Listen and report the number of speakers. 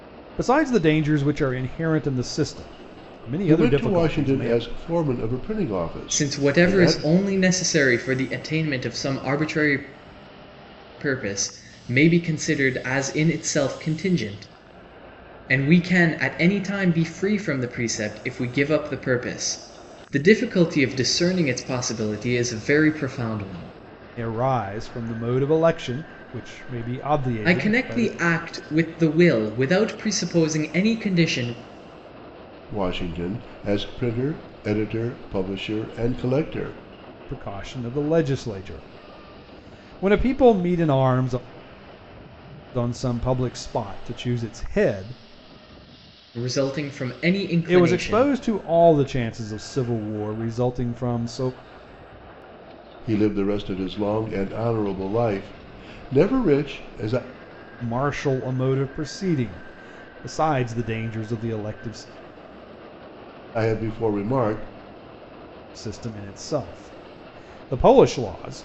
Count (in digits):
3